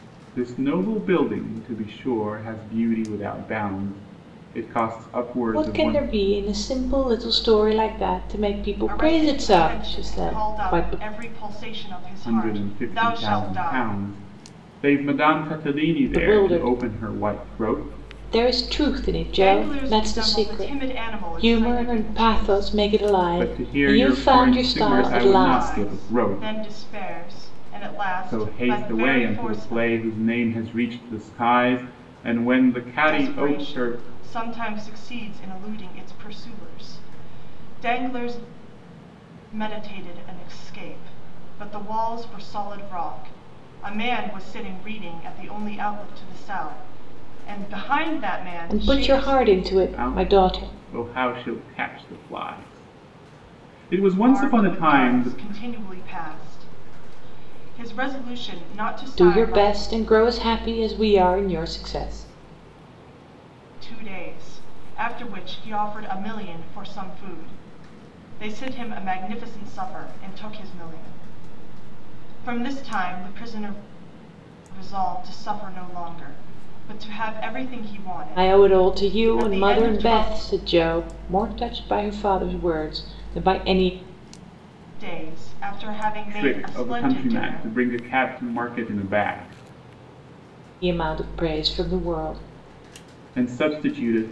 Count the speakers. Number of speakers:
3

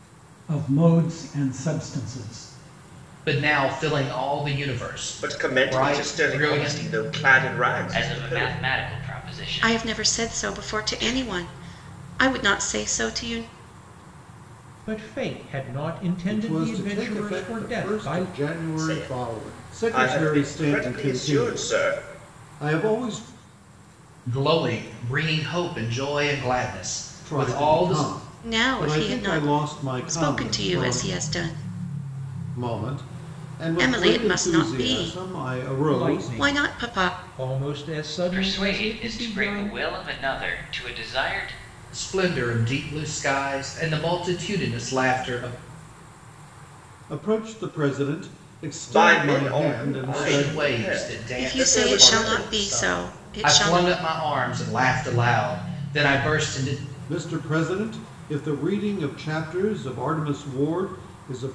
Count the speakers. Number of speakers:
7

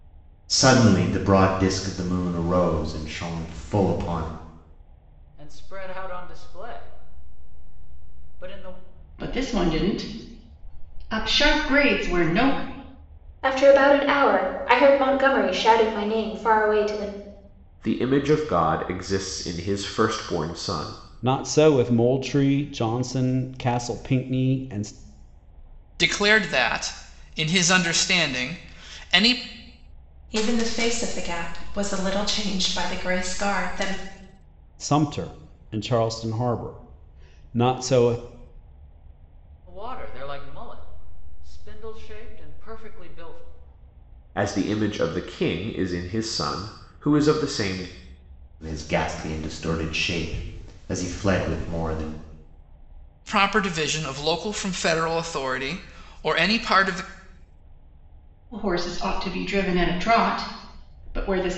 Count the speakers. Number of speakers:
8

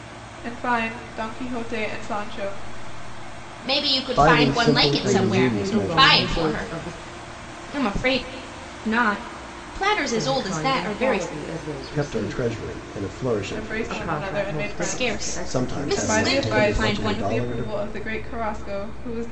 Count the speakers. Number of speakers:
4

